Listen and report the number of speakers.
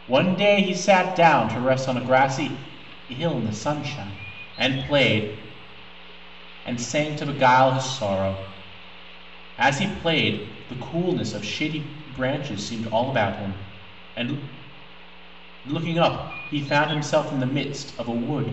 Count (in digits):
1